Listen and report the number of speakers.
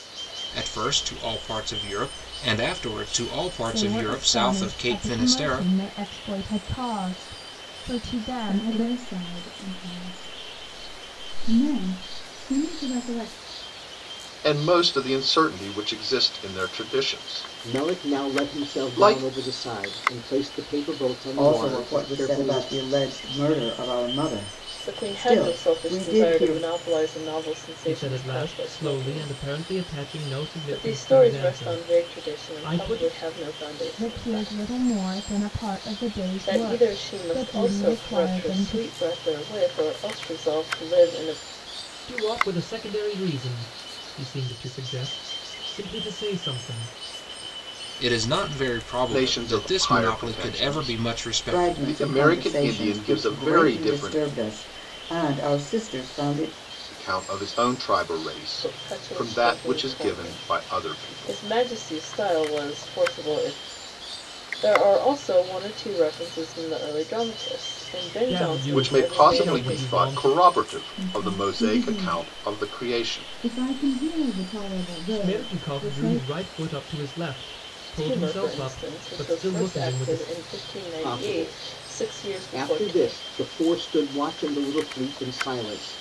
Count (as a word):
eight